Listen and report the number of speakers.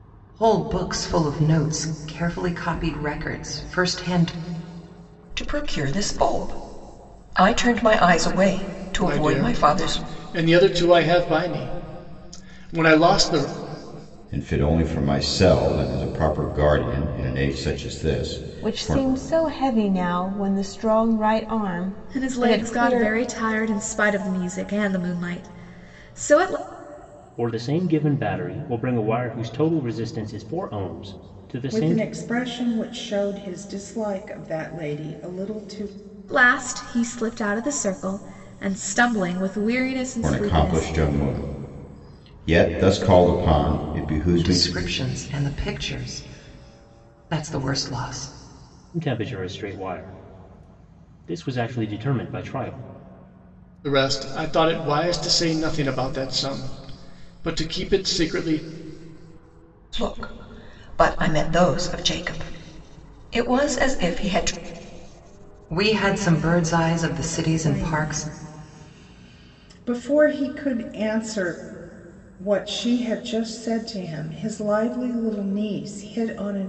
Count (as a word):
eight